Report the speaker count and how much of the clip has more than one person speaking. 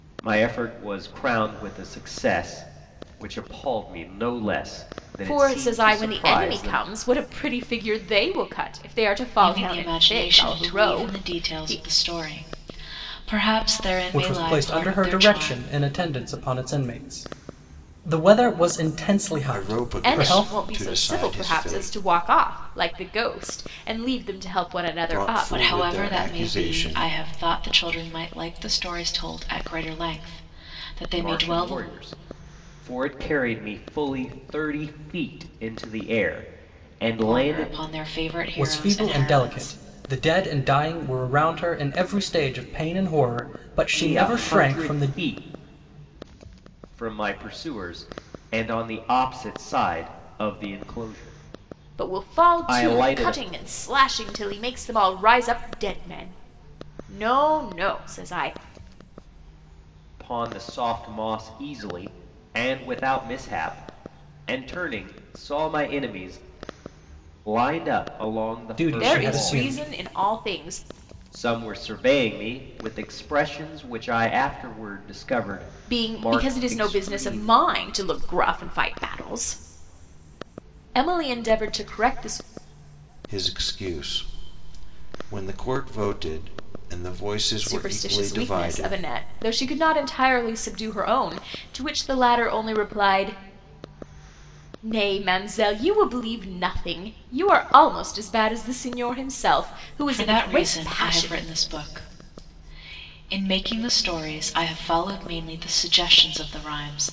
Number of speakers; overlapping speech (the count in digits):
5, about 20%